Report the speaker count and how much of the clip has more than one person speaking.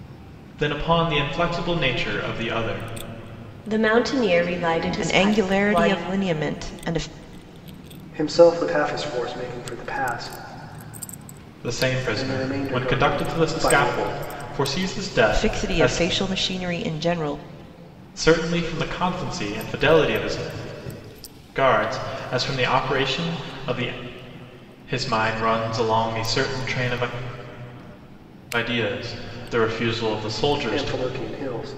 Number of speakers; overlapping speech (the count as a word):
four, about 12%